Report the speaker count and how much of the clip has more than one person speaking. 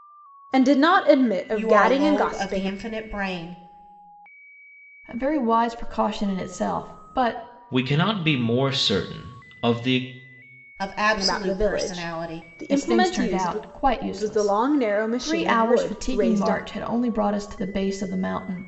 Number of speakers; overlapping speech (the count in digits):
4, about 29%